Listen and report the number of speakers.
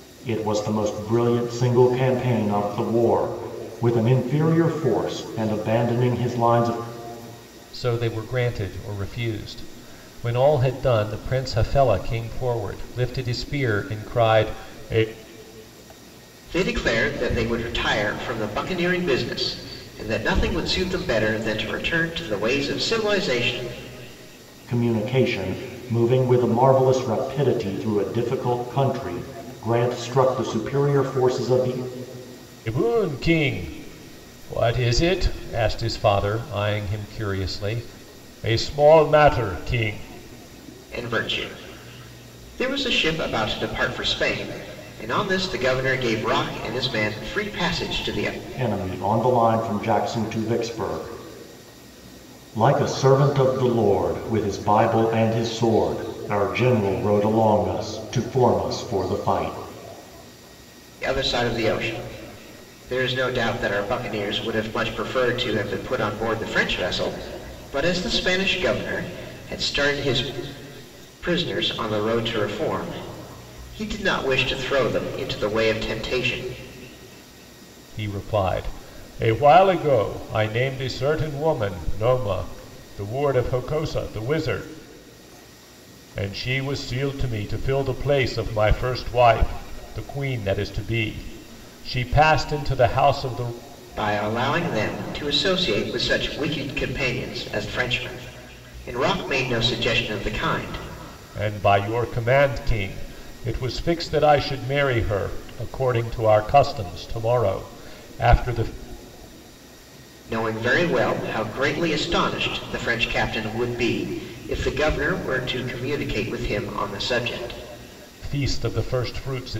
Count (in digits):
3